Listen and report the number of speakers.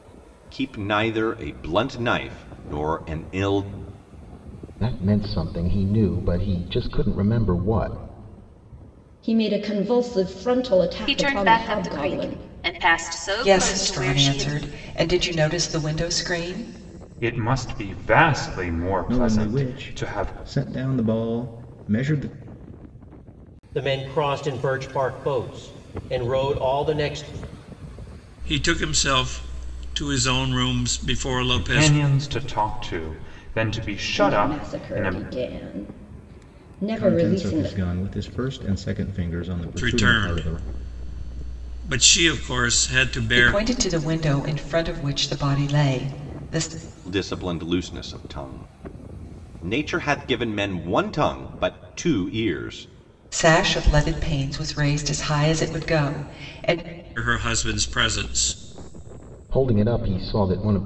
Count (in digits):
9